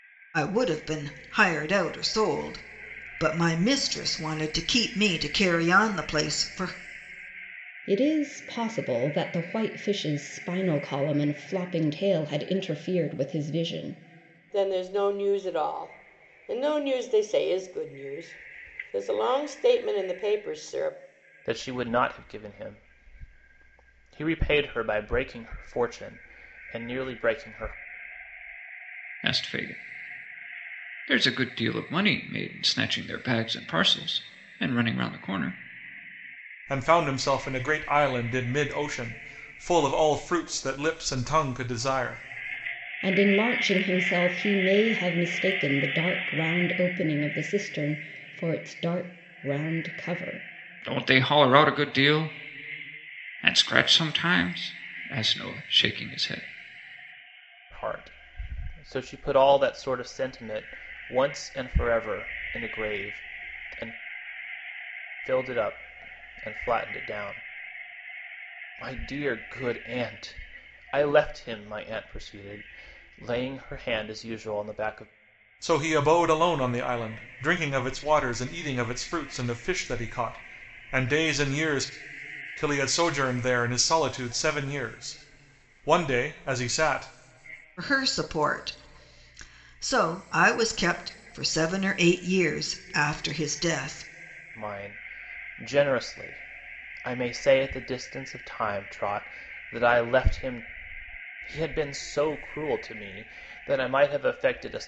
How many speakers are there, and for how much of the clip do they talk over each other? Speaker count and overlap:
6, no overlap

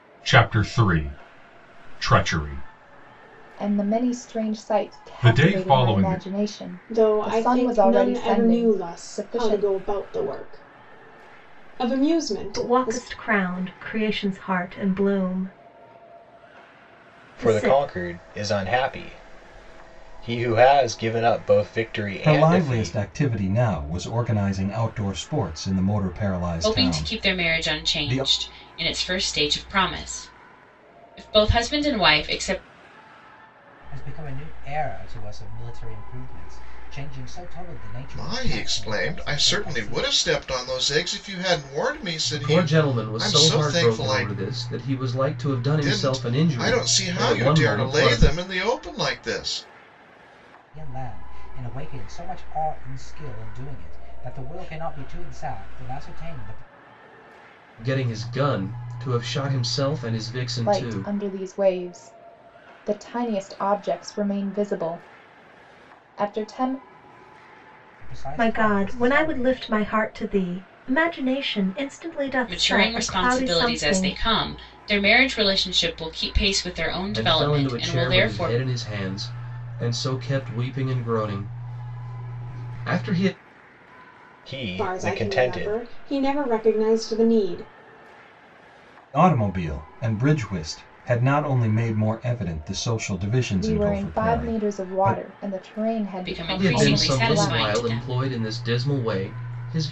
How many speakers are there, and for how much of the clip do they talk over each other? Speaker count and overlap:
10, about 26%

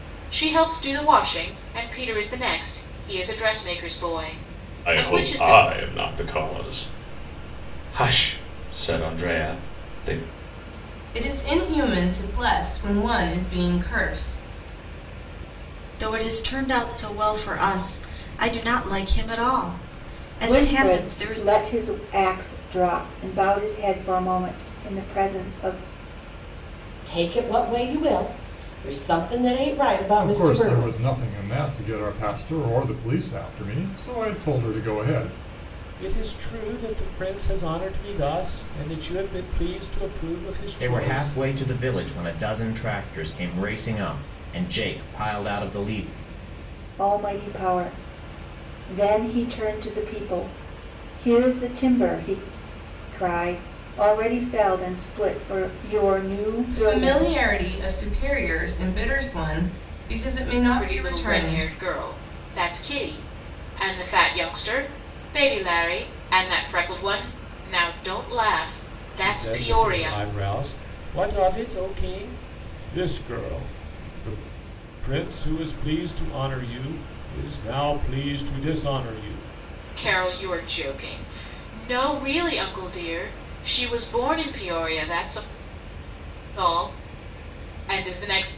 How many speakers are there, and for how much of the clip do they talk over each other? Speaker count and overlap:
9, about 7%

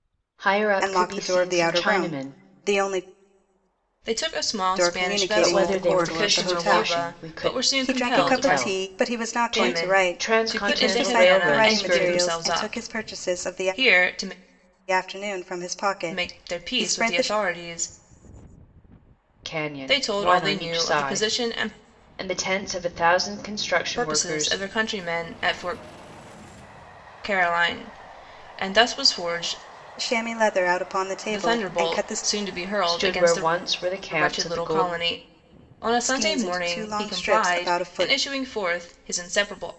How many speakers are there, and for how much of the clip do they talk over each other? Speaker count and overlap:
3, about 47%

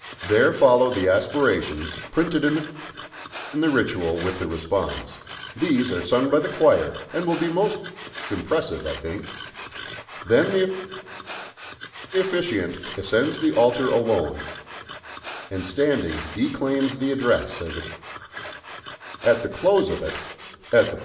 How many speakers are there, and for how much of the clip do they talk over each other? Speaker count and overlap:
1, no overlap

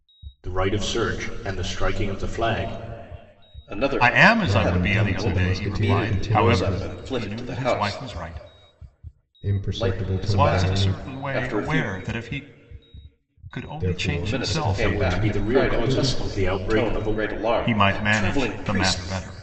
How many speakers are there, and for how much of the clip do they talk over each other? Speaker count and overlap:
4, about 57%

